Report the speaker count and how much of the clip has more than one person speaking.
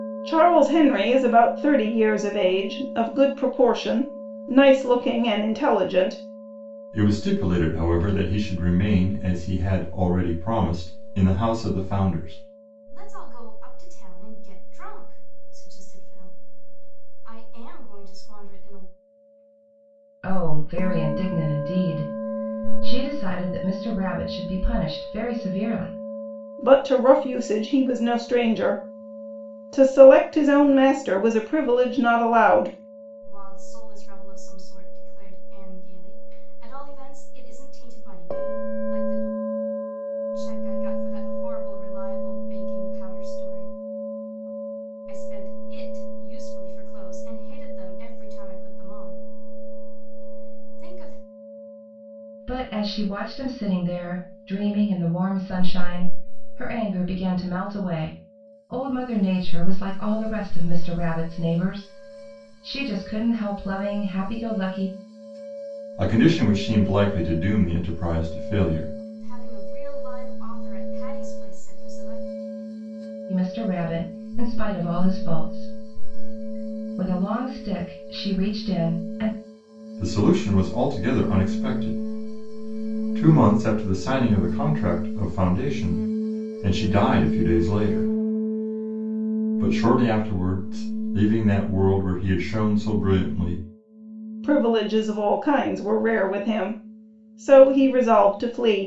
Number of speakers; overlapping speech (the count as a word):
four, no overlap